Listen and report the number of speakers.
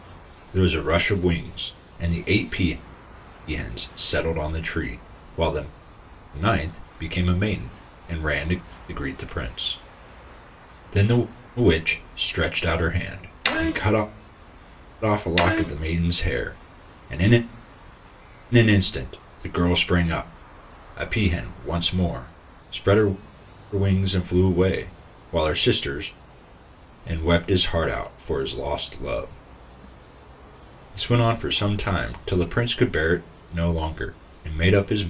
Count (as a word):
one